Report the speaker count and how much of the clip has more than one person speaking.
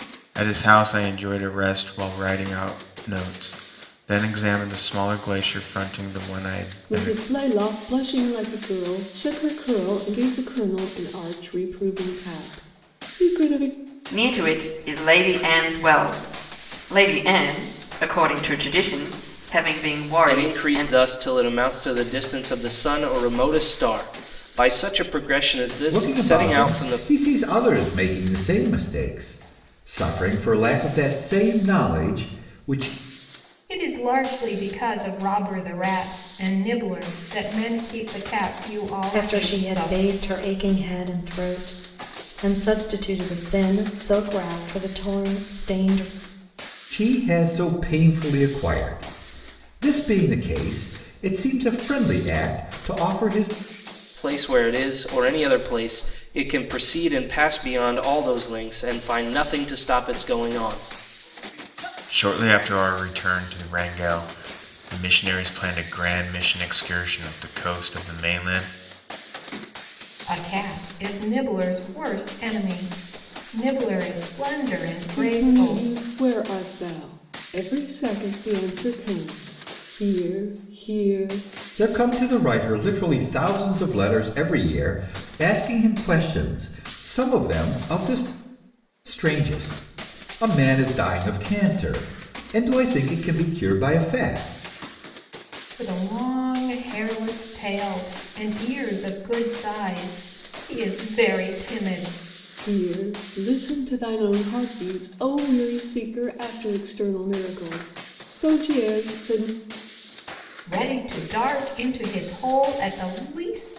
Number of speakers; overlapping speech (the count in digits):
7, about 3%